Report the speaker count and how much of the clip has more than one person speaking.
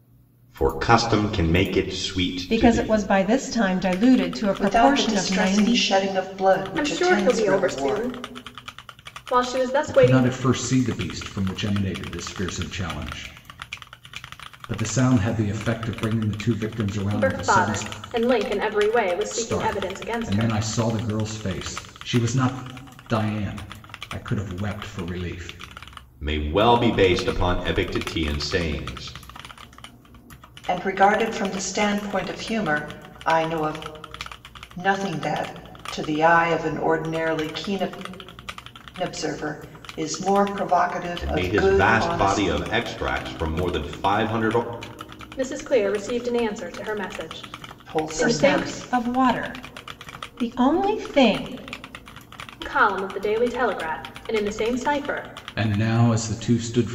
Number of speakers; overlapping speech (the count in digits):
5, about 14%